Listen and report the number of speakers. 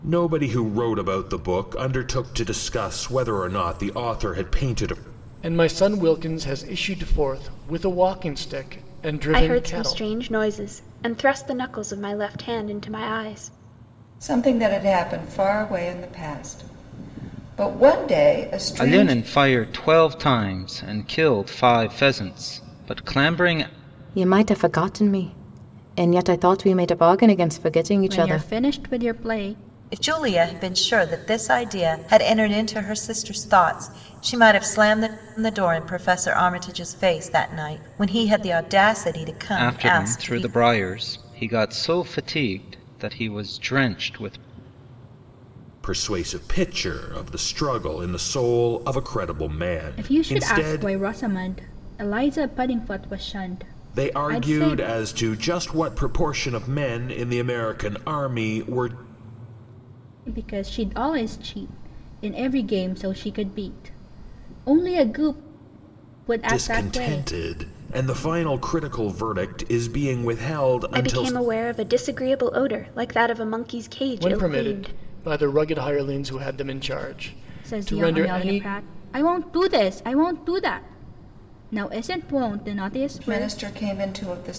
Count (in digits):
8